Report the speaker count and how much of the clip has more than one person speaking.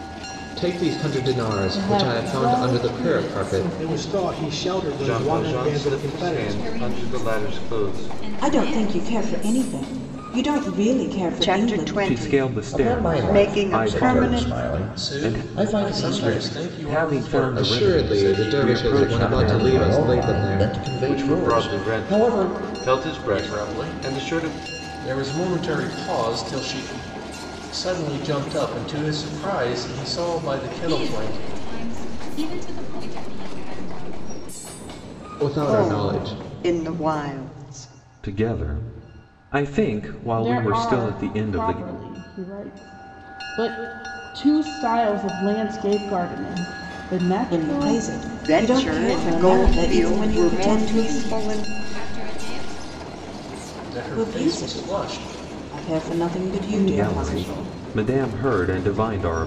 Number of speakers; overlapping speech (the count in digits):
10, about 47%